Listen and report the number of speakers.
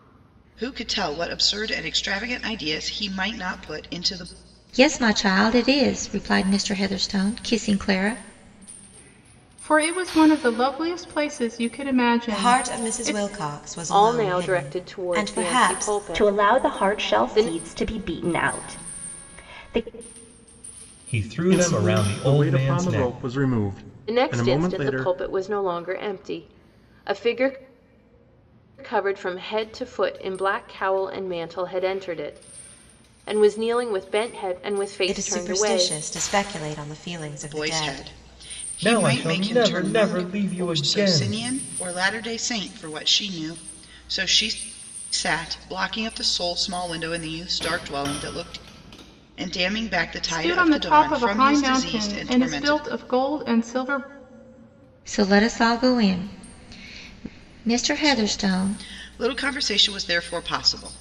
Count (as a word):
eight